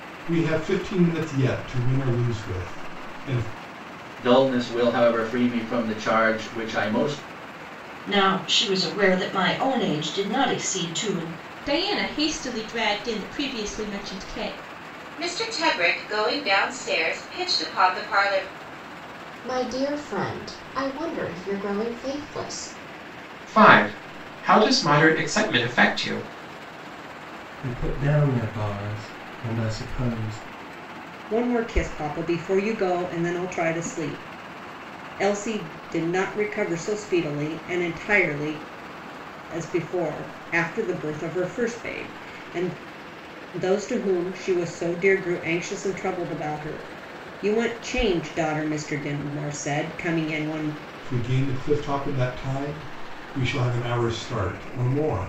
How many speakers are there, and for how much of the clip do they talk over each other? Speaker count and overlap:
nine, no overlap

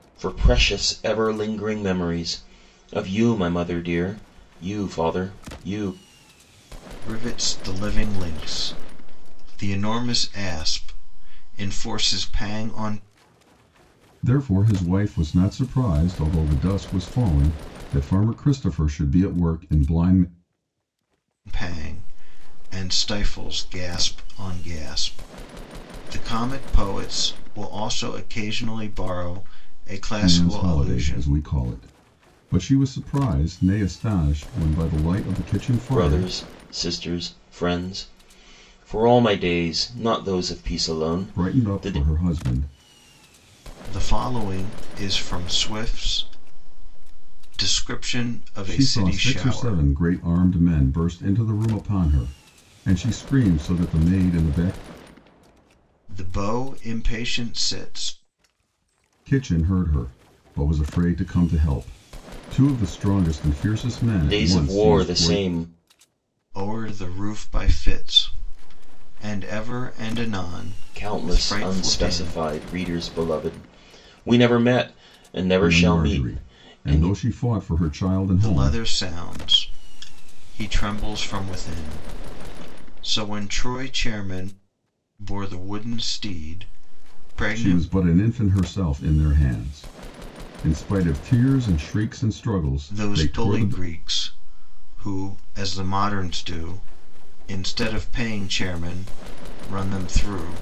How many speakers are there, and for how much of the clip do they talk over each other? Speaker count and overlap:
three, about 9%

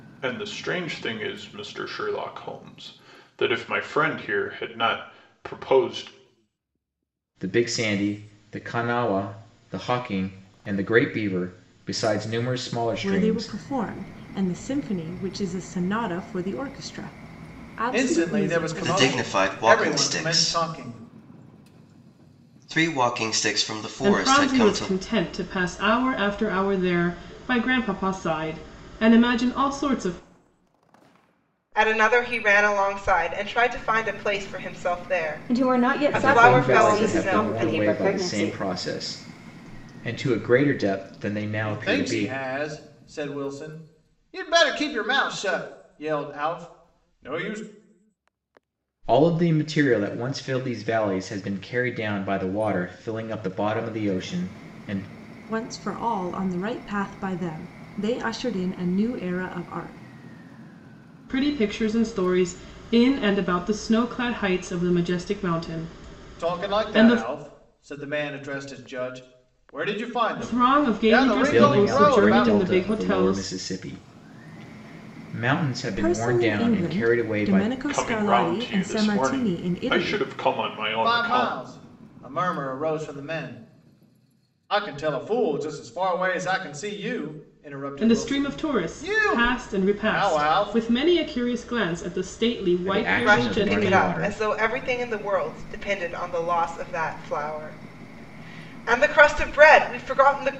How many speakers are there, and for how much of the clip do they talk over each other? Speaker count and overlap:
eight, about 22%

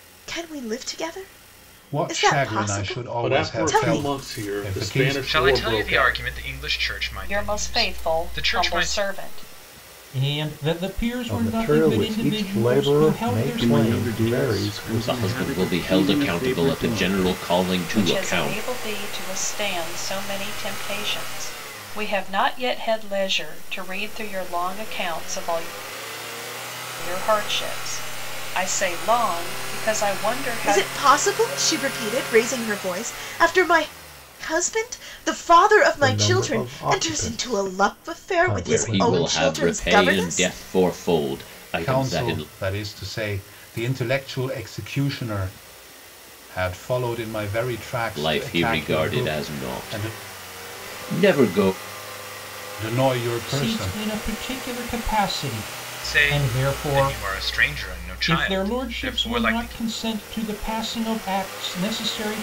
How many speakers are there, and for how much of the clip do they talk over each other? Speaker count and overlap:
nine, about 39%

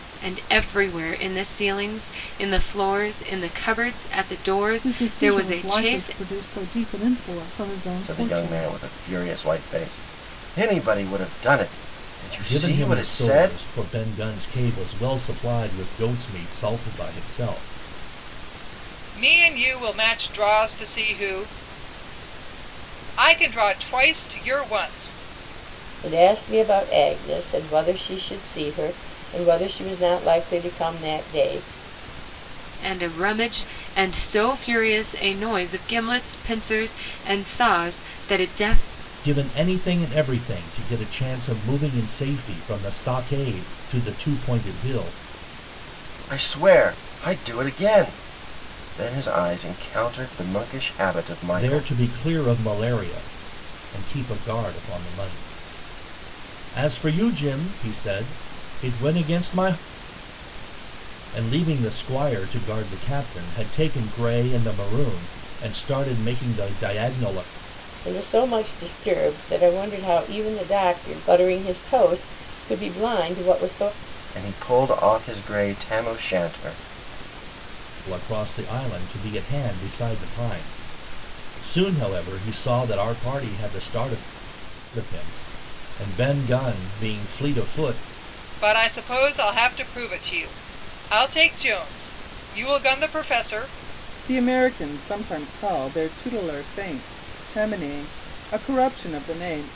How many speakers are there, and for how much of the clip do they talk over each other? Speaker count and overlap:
six, about 4%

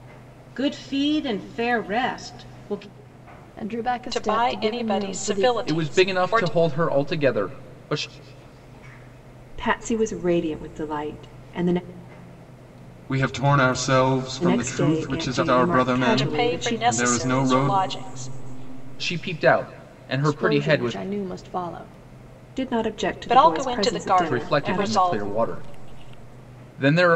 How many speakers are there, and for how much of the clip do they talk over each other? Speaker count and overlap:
six, about 32%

